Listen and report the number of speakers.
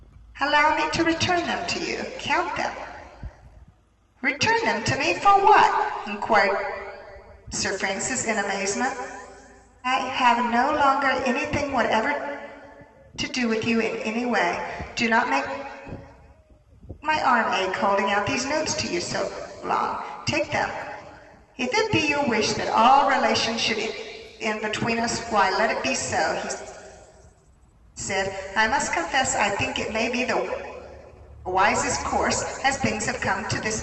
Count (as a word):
one